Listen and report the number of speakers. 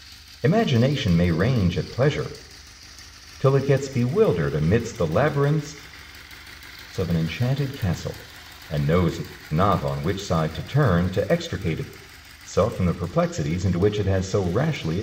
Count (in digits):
1